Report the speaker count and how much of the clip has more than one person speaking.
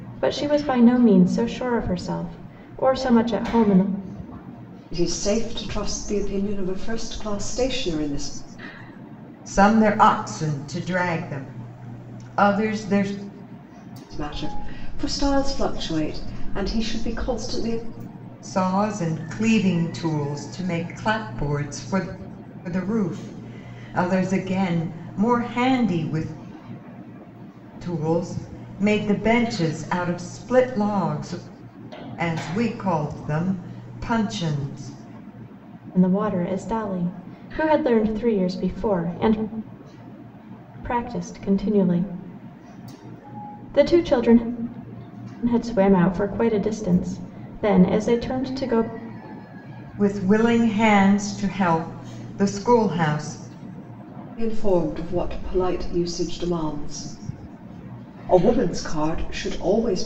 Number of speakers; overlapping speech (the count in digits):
3, no overlap